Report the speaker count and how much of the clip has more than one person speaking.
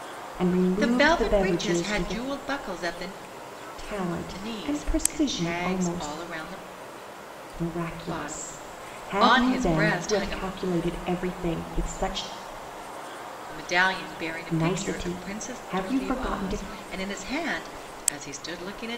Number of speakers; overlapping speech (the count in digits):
2, about 42%